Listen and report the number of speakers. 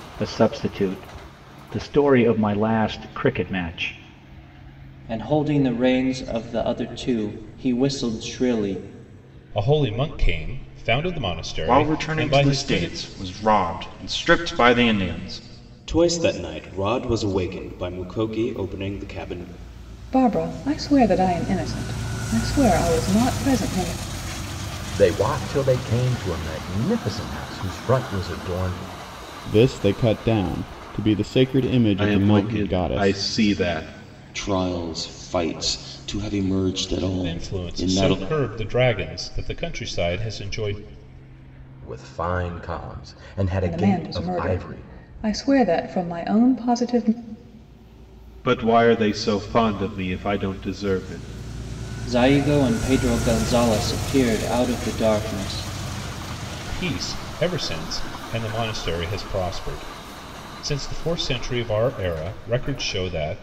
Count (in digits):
10